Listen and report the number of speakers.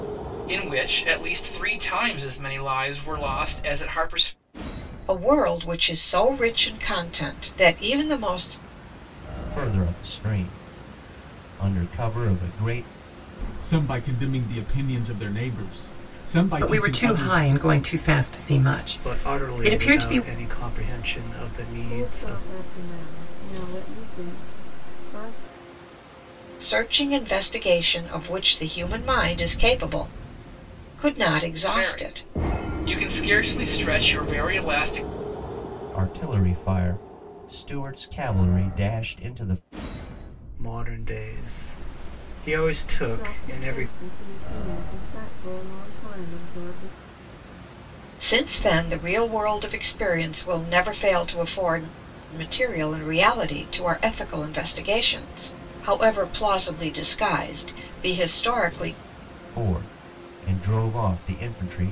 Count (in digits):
7